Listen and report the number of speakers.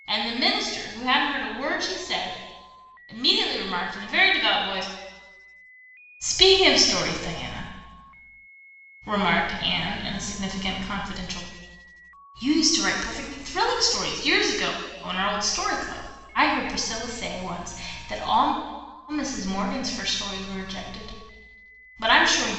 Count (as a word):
one